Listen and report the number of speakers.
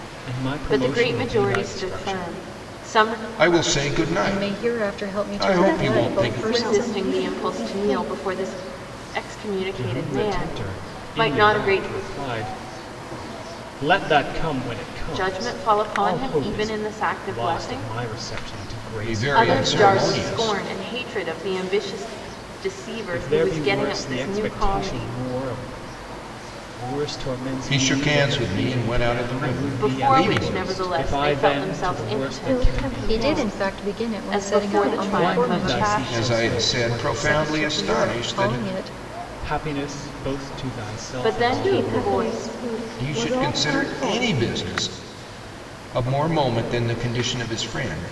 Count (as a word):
five